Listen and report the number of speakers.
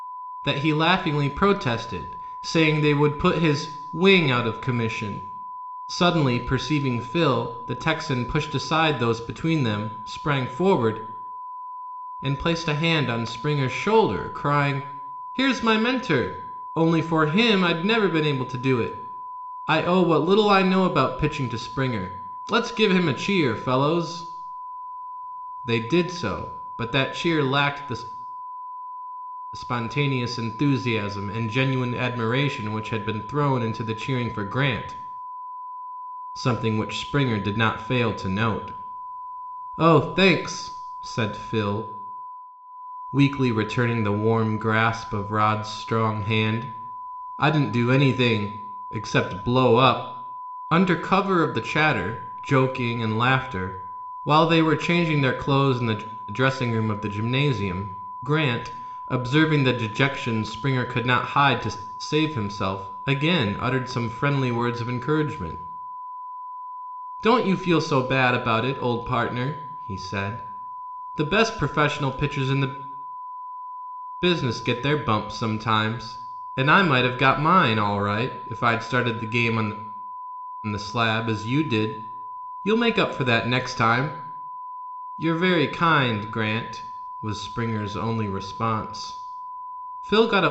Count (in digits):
1